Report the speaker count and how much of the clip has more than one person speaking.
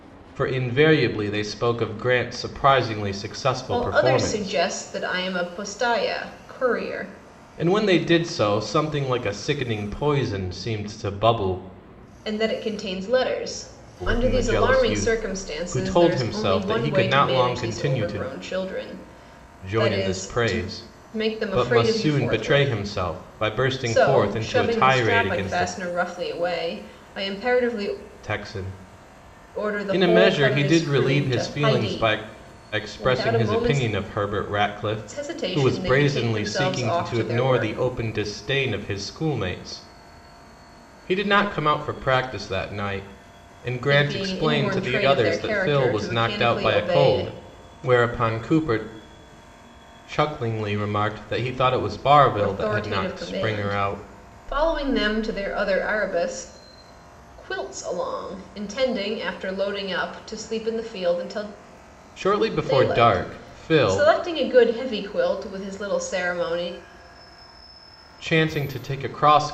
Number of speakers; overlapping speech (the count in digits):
2, about 33%